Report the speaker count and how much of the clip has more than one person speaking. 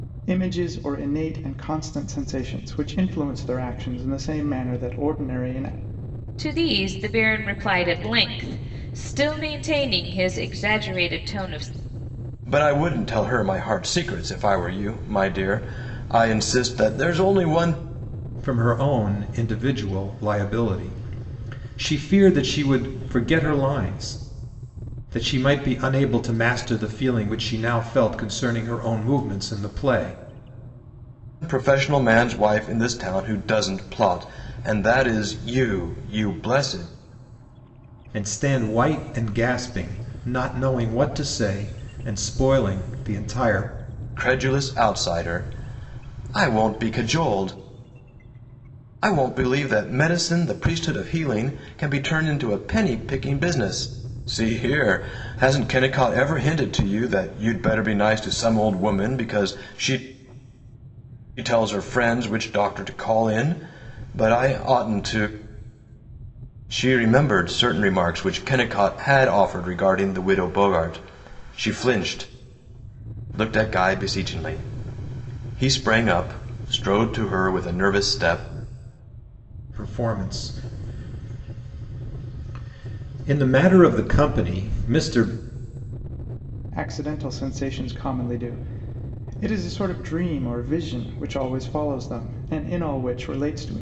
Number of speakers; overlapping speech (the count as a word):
four, no overlap